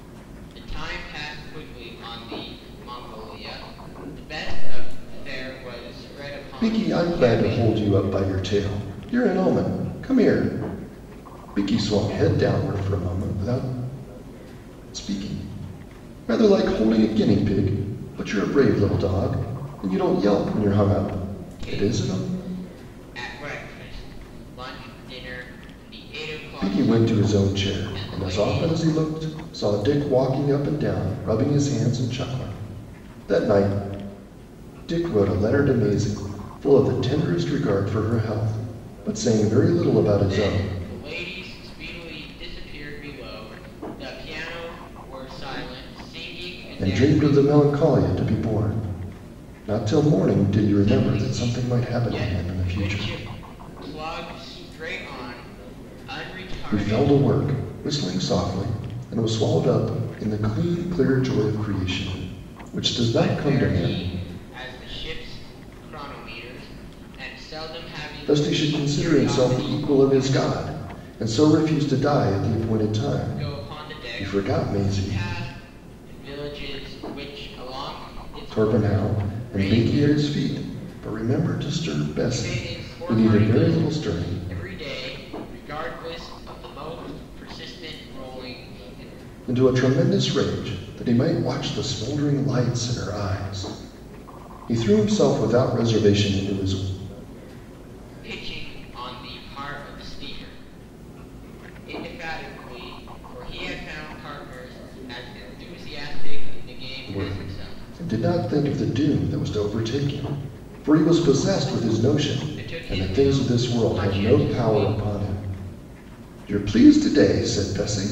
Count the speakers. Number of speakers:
2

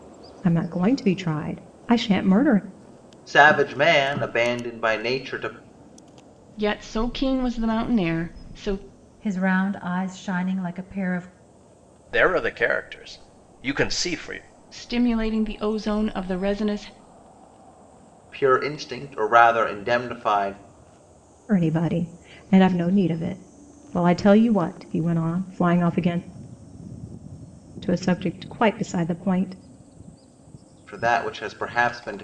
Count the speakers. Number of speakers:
5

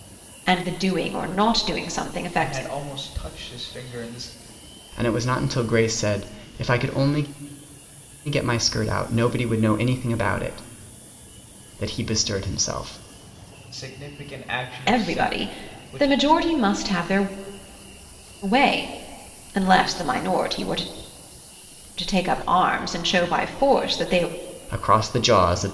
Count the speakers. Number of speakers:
3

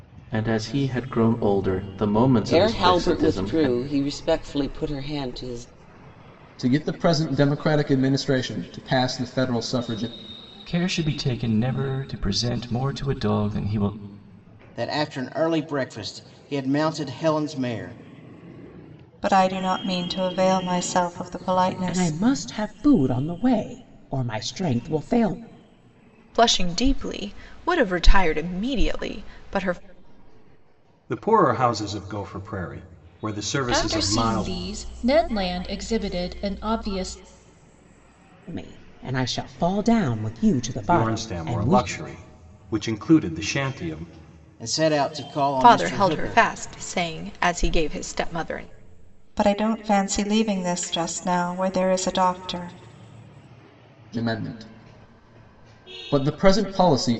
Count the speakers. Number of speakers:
10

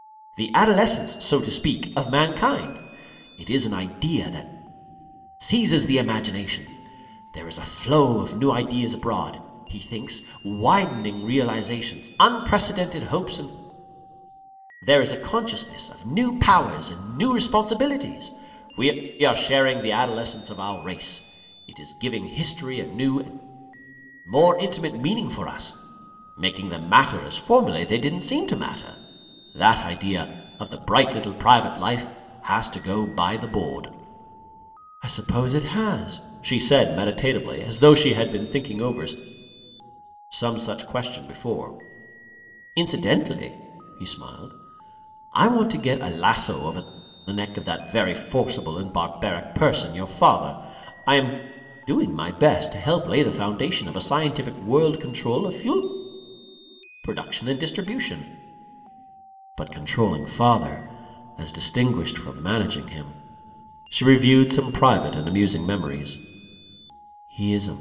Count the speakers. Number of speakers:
1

